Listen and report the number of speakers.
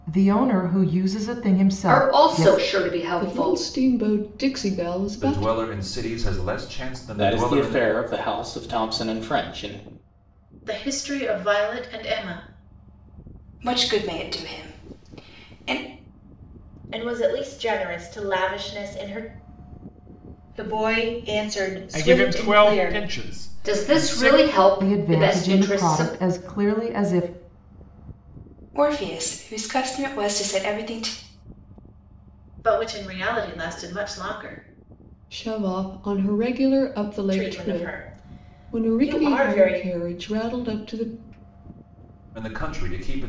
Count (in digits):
10